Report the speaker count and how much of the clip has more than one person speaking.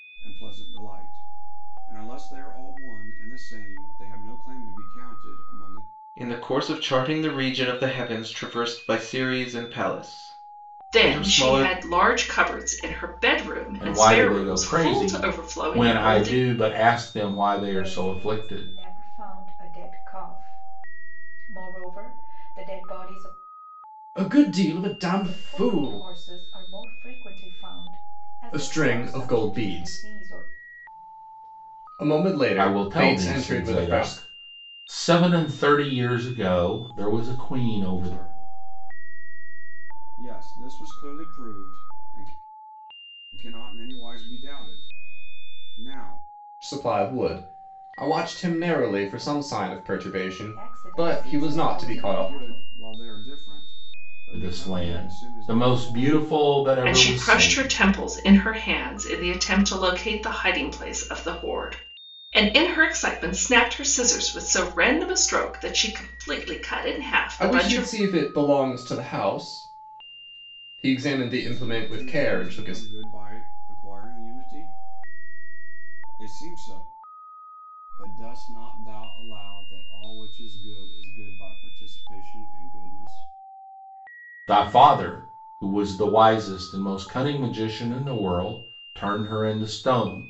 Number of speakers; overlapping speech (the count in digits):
6, about 19%